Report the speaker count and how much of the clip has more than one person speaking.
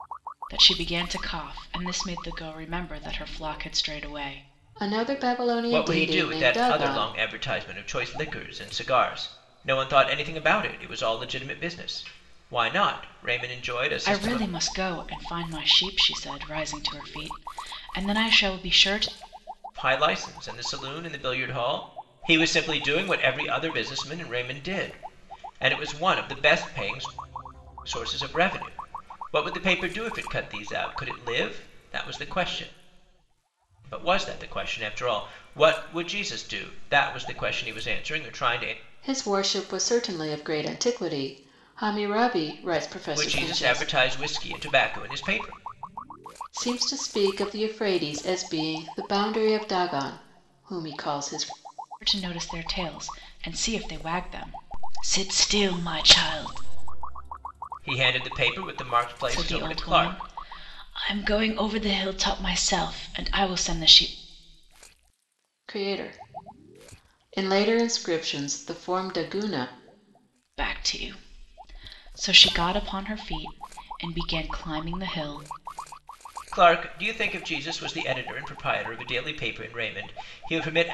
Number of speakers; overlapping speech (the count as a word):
three, about 5%